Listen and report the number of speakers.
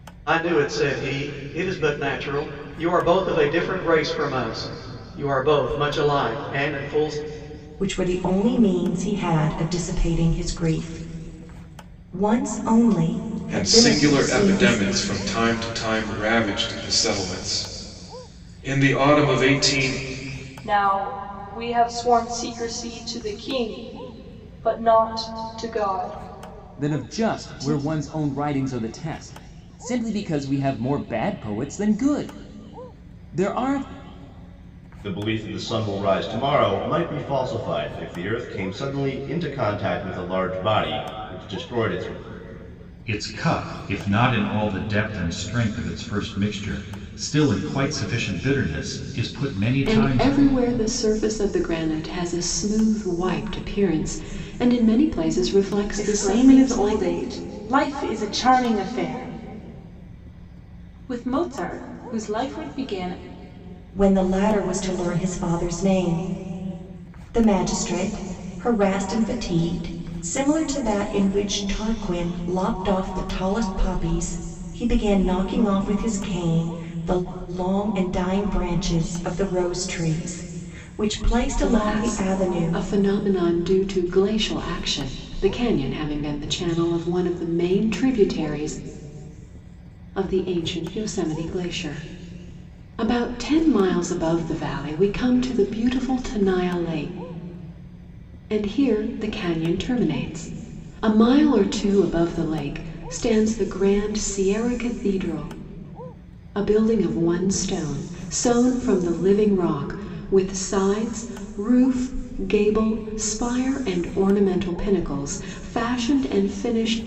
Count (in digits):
9